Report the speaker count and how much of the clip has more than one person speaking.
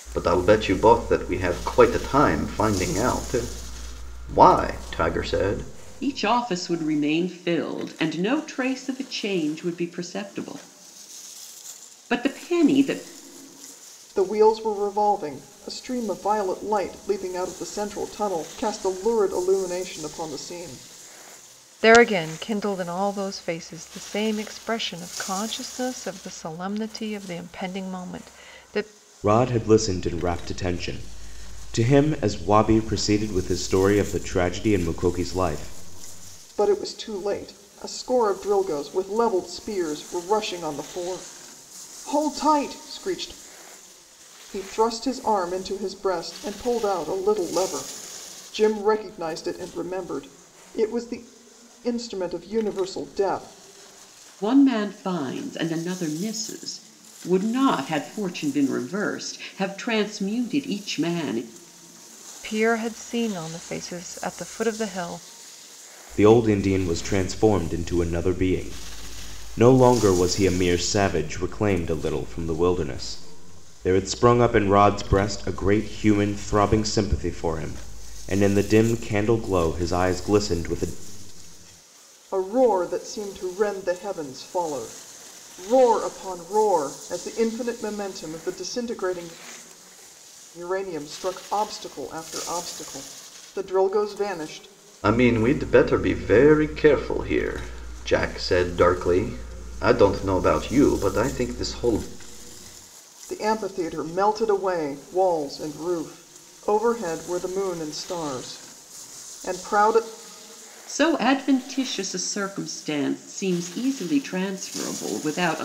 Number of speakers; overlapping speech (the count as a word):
five, no overlap